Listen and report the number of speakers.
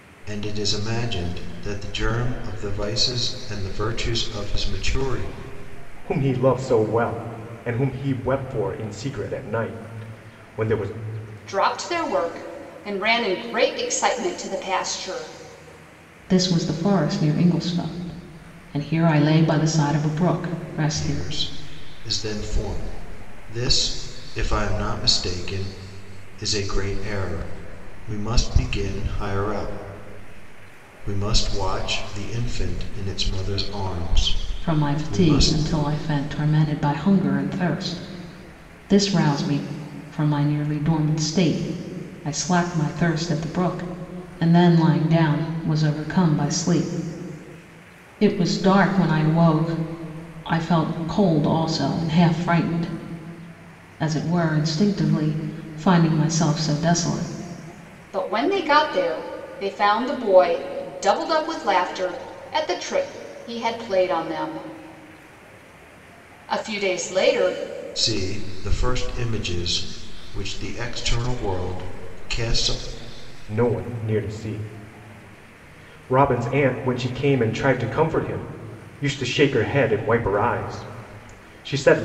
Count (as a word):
four